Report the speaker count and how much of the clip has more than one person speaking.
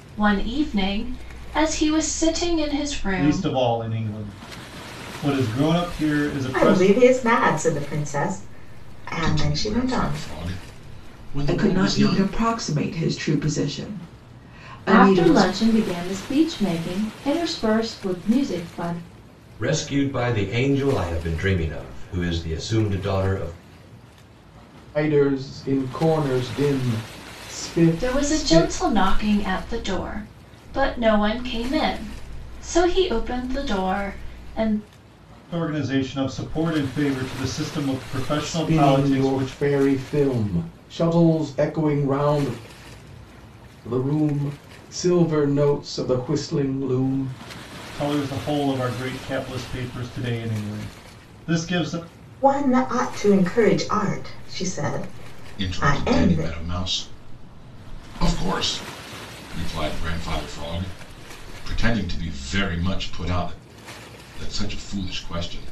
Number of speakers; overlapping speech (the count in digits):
8, about 9%